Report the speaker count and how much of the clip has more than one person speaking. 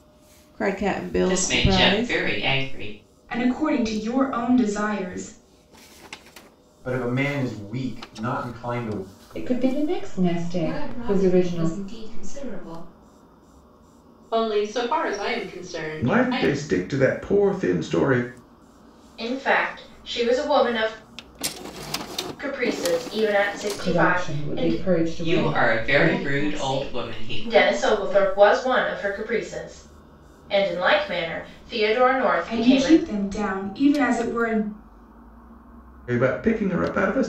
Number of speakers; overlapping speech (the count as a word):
nine, about 20%